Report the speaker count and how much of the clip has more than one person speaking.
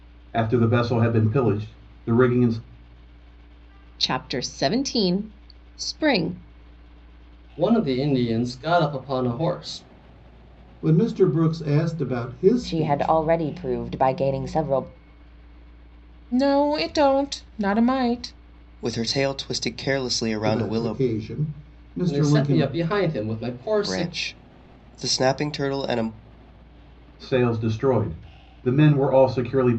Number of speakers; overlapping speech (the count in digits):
7, about 8%